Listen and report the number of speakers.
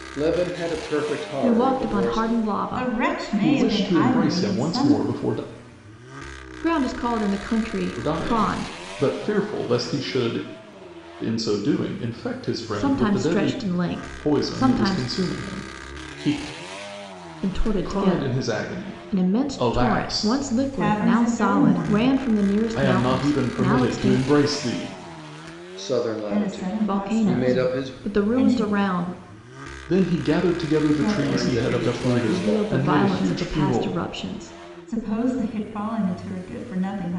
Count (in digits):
4